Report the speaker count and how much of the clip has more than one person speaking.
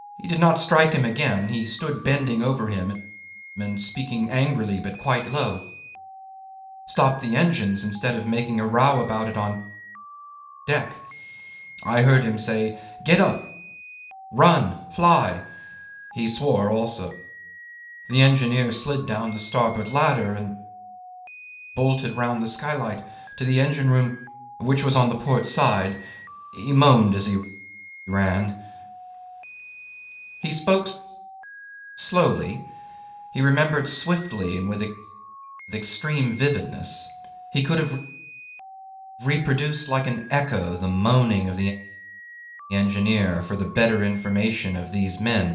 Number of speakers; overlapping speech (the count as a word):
one, no overlap